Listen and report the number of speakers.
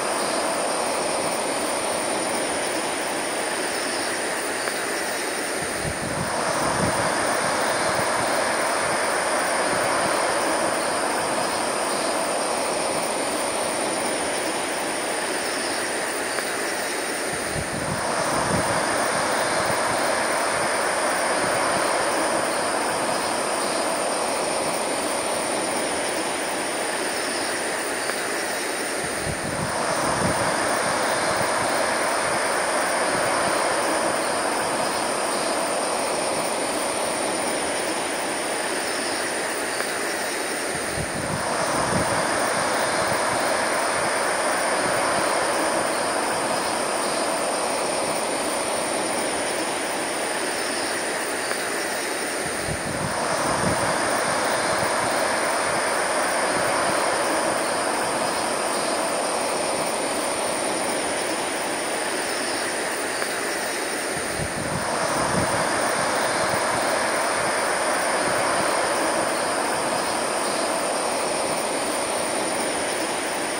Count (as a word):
zero